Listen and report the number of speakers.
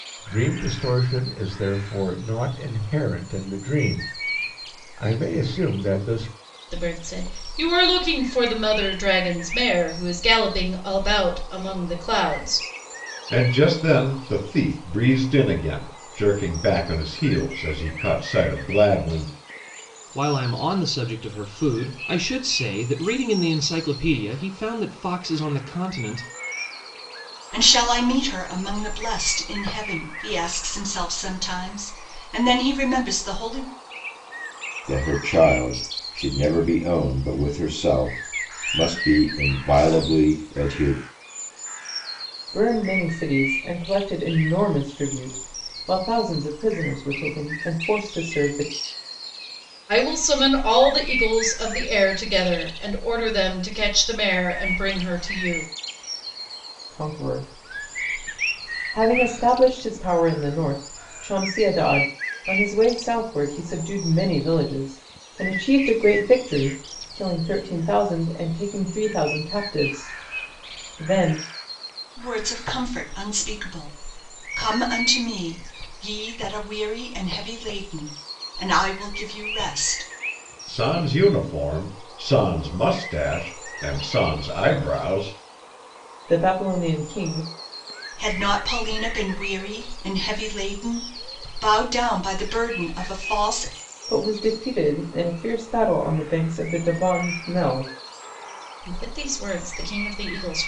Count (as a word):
seven